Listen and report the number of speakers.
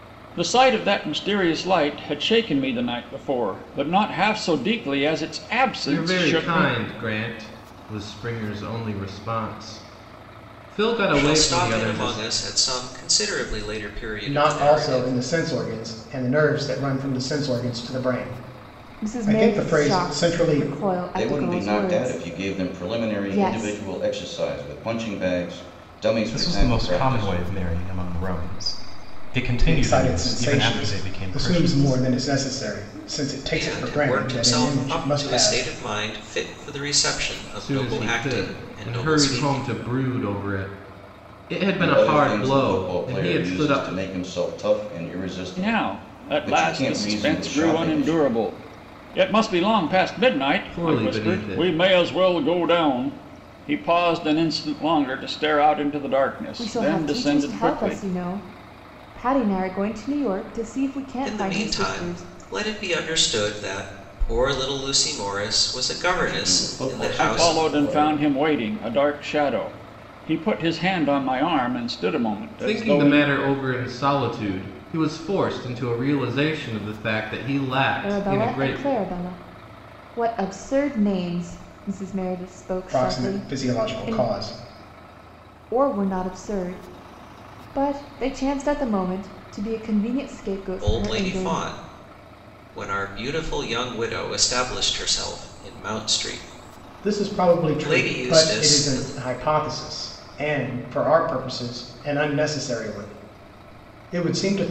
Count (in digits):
7